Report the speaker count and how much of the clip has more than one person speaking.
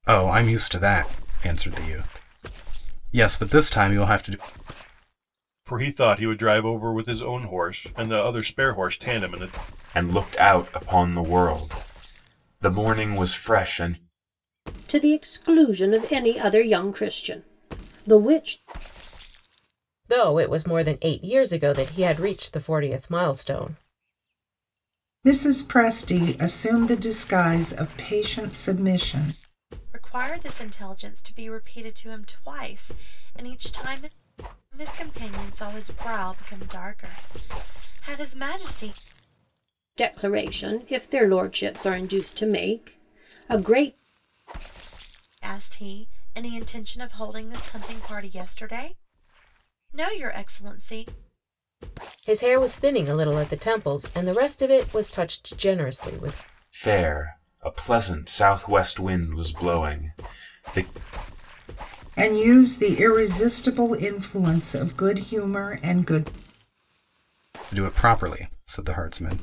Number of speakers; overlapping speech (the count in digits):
7, no overlap